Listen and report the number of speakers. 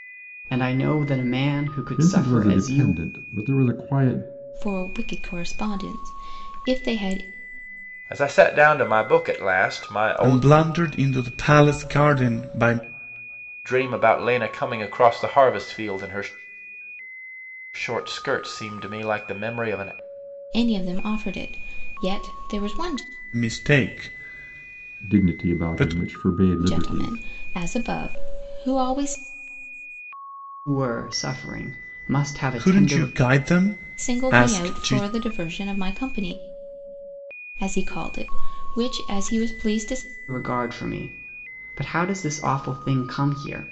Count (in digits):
5